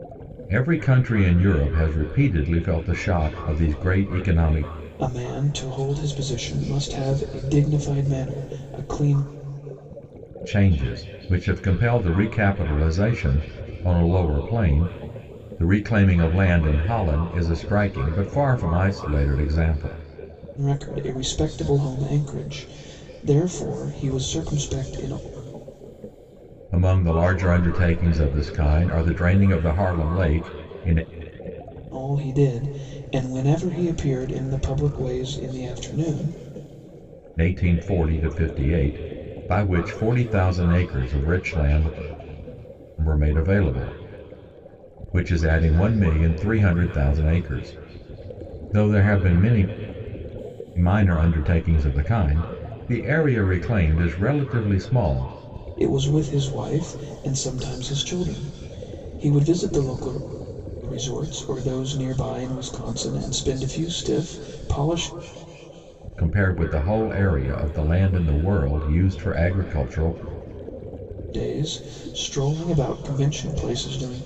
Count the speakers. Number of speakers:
two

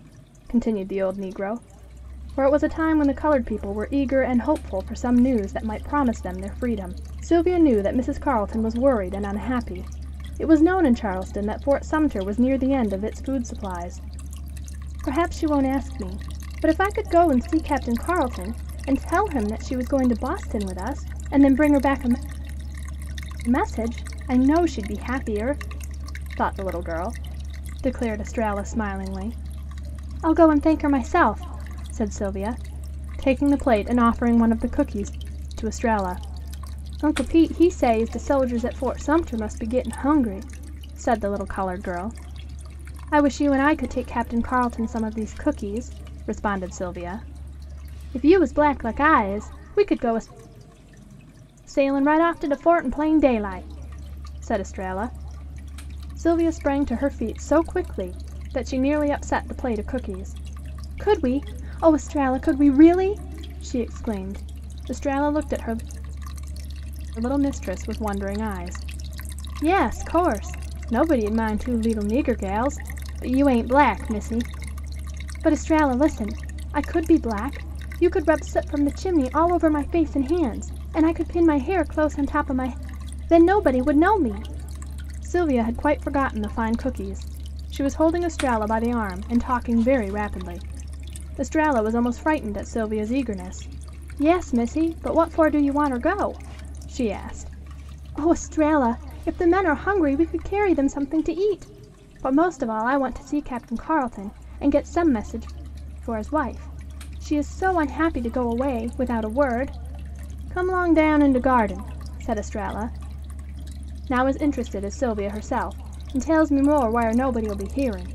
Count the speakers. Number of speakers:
one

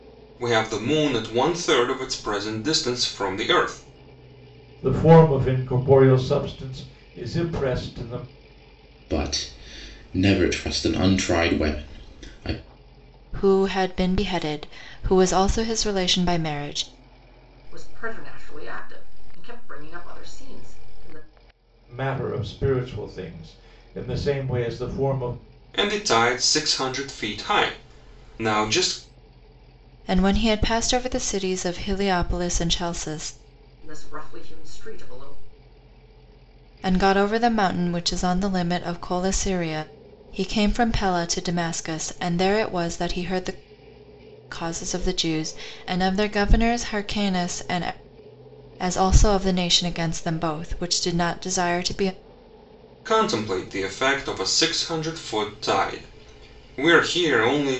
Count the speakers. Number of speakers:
five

